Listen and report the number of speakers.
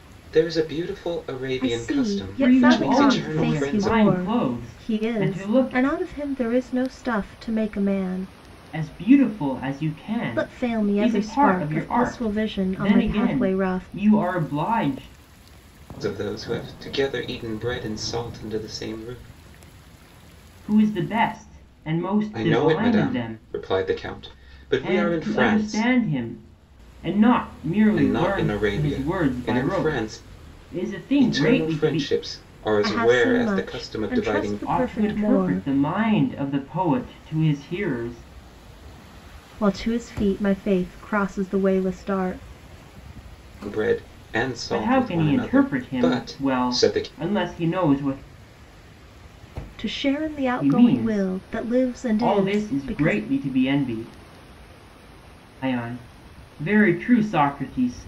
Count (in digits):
3